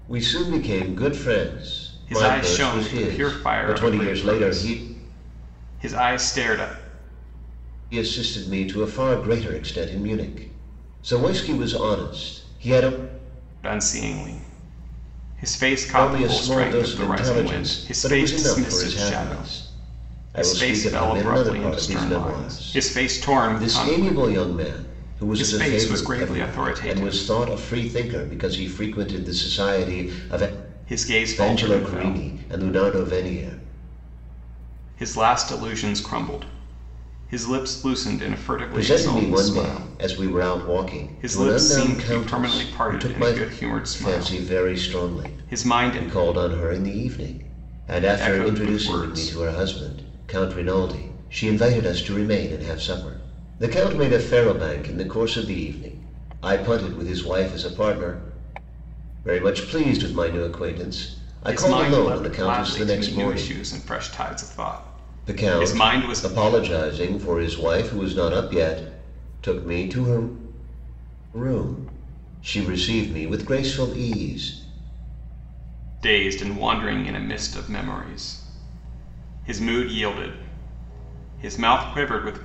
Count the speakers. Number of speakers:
2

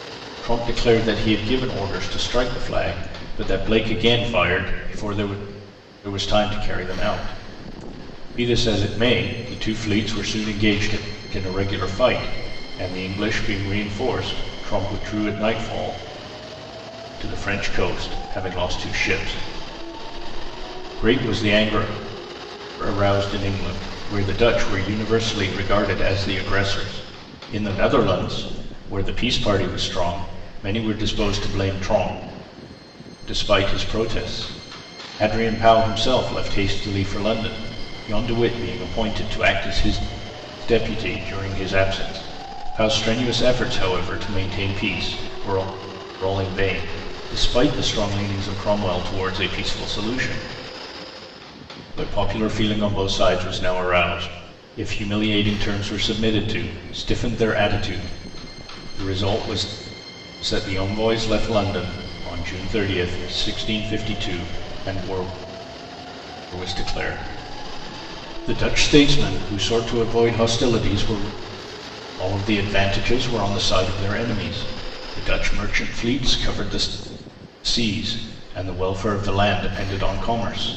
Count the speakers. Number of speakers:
1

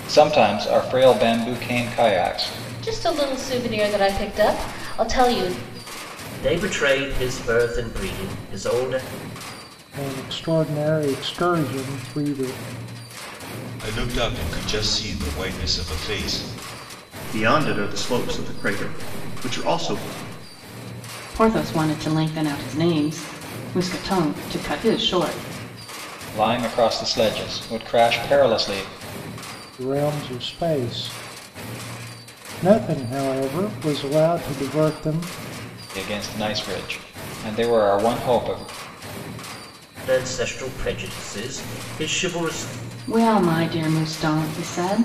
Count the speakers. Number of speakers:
7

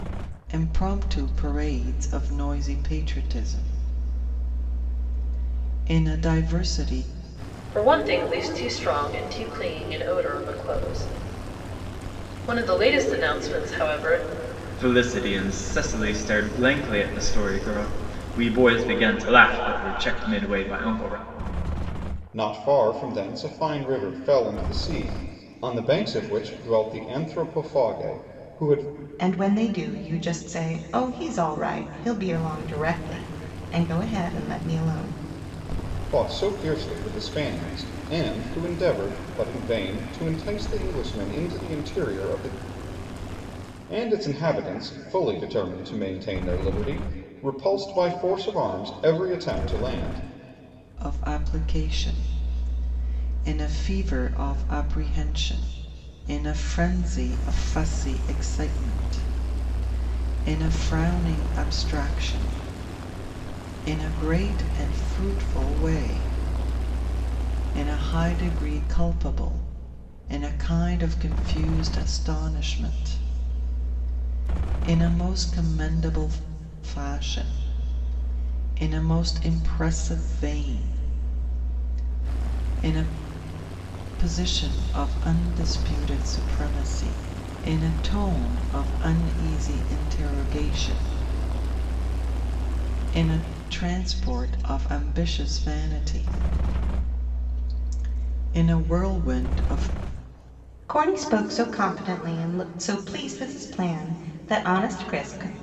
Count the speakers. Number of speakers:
5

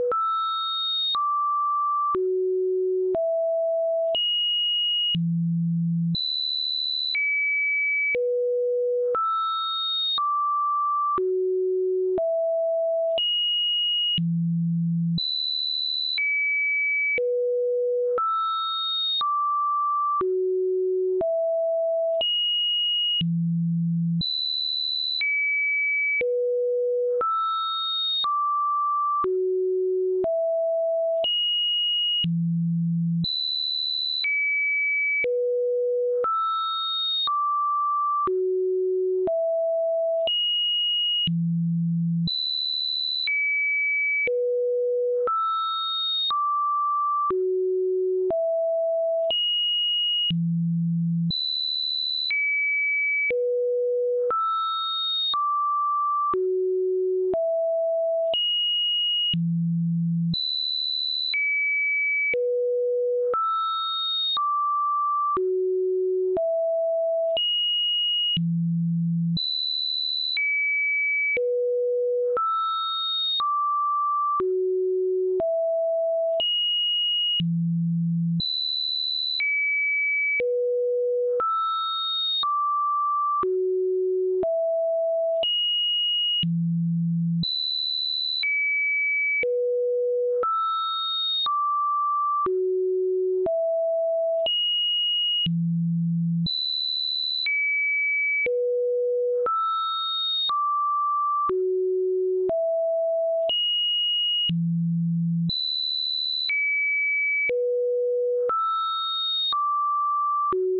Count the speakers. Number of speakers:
0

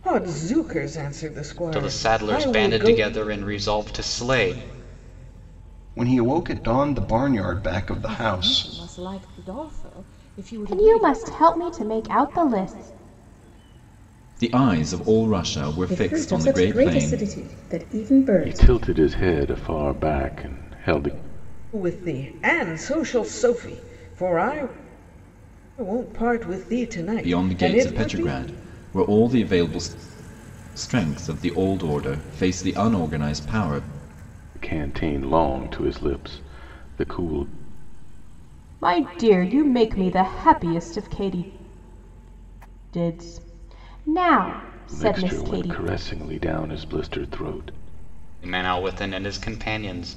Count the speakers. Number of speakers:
8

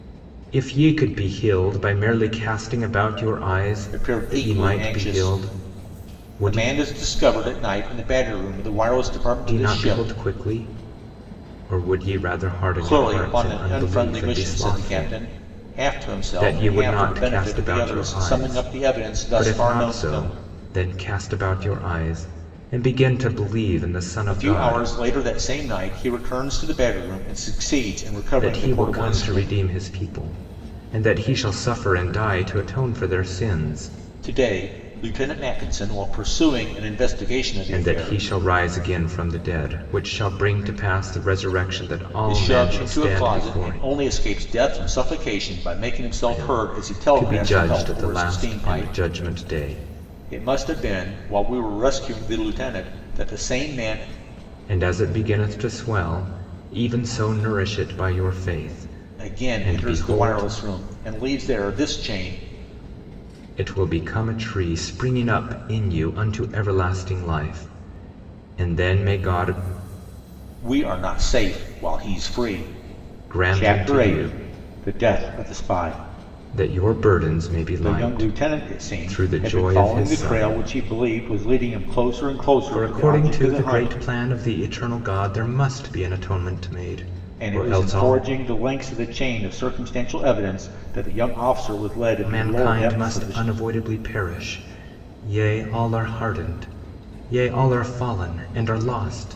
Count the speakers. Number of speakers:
2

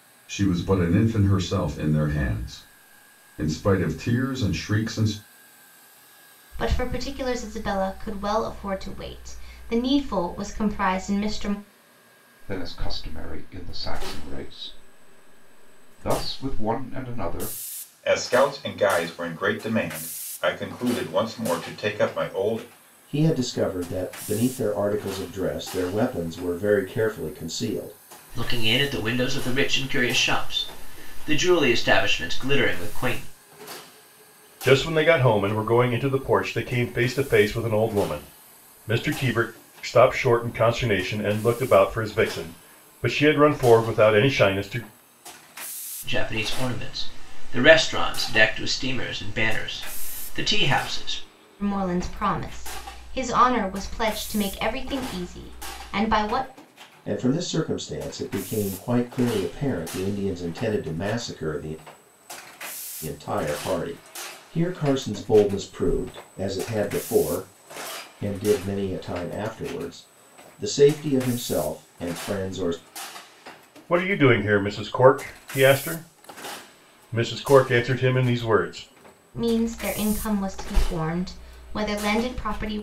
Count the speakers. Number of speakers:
7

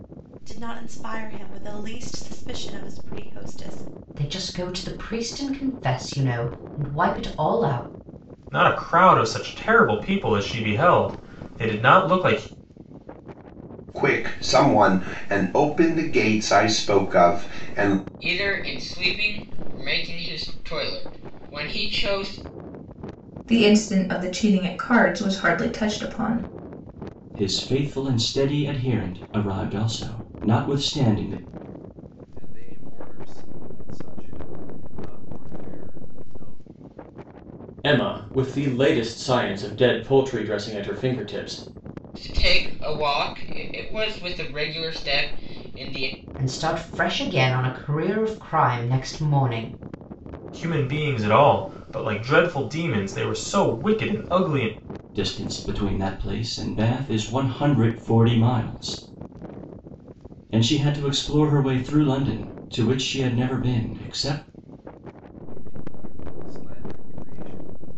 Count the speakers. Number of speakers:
9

